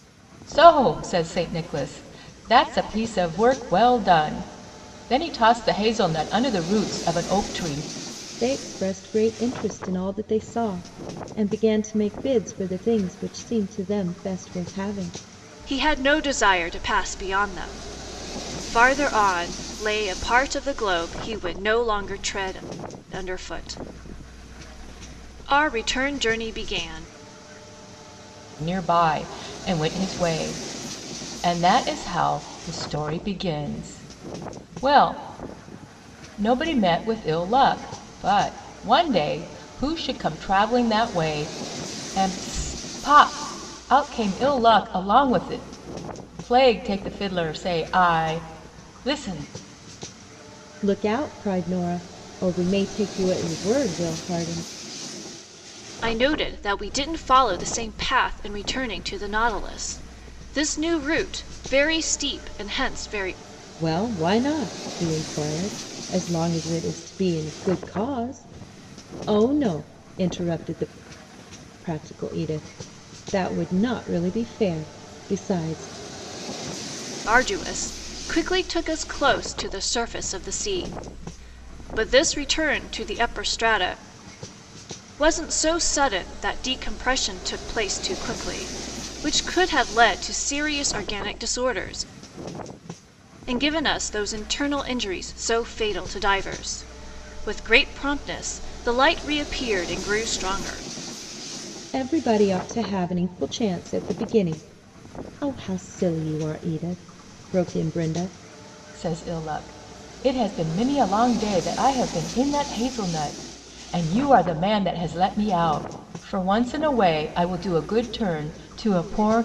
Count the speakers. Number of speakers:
three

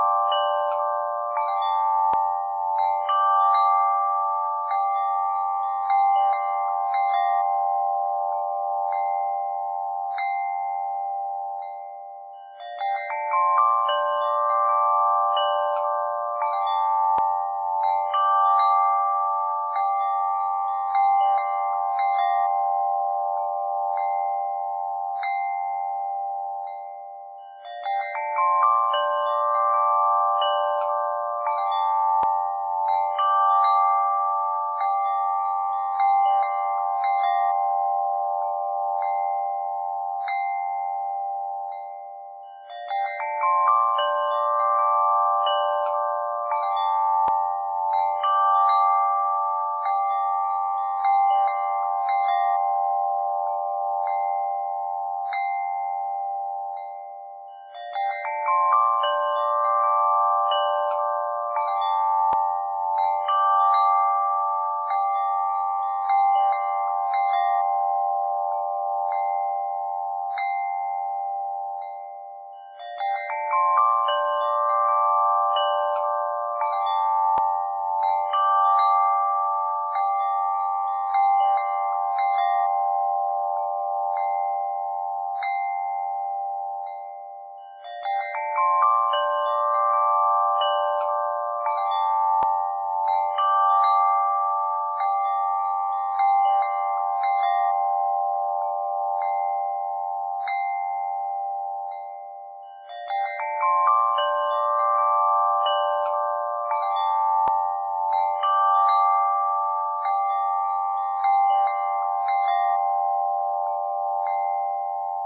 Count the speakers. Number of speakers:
zero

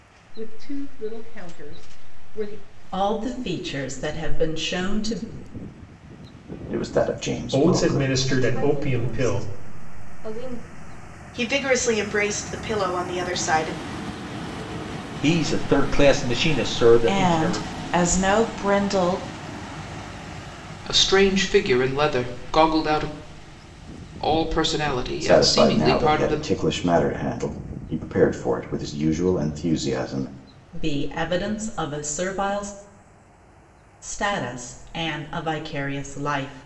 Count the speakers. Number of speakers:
nine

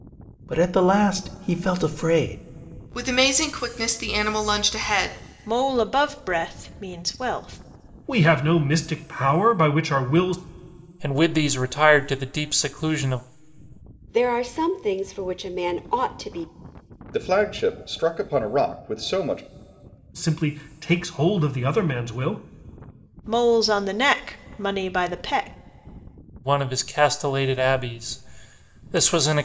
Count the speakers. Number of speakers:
seven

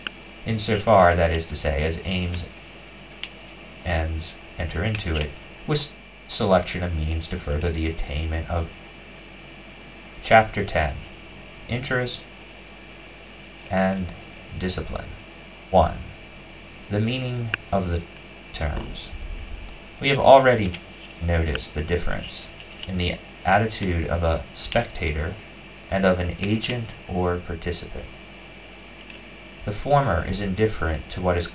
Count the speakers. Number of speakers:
one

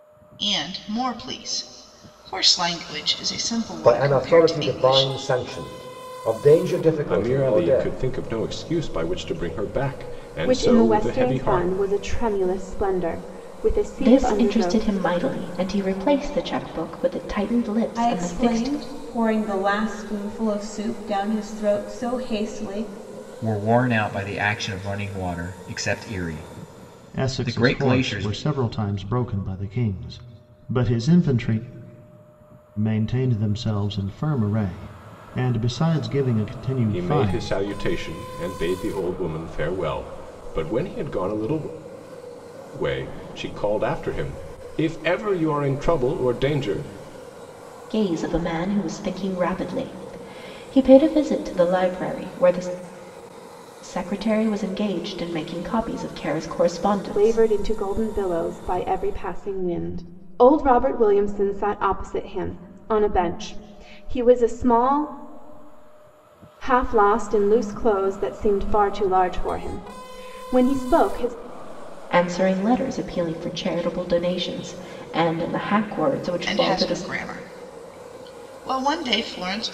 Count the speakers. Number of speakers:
eight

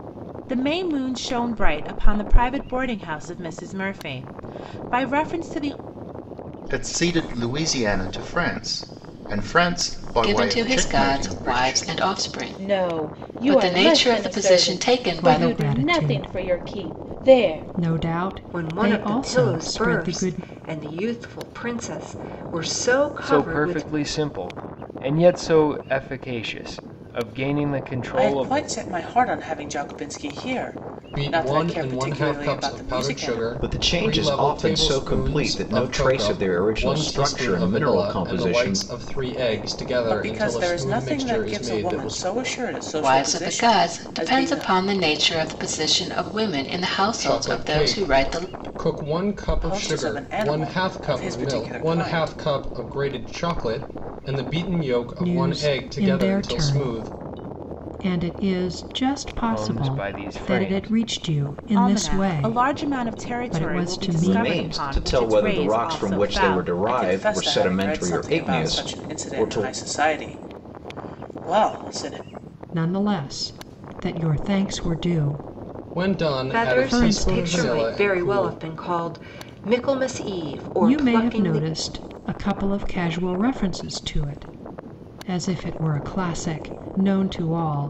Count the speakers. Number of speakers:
ten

